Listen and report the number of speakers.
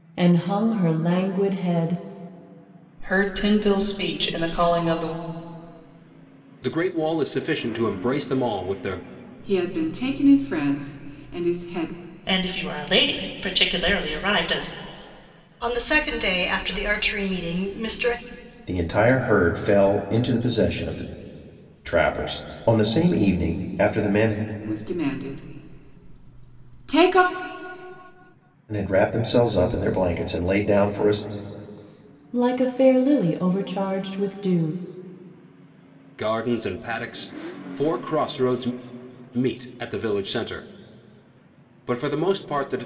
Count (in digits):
7